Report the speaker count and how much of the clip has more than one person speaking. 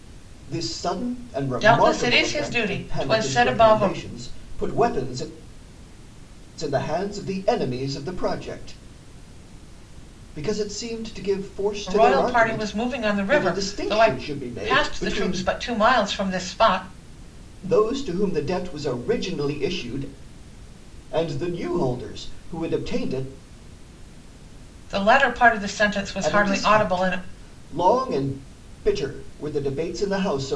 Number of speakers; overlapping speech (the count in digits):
2, about 20%